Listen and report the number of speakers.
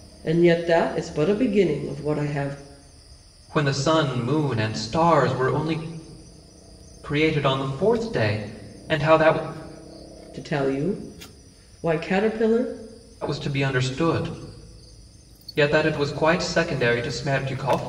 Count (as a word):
two